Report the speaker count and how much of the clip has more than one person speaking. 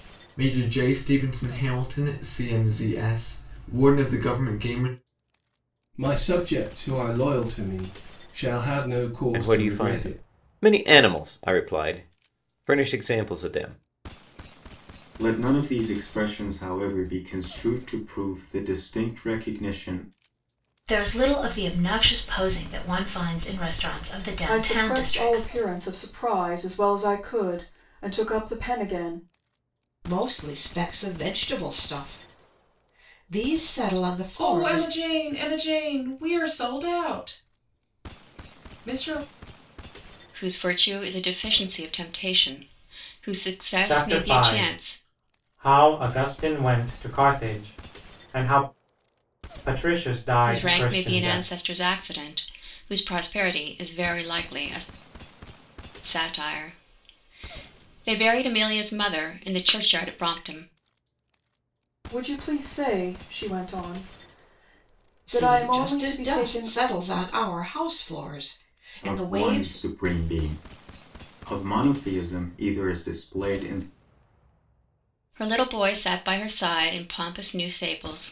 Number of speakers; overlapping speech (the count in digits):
10, about 9%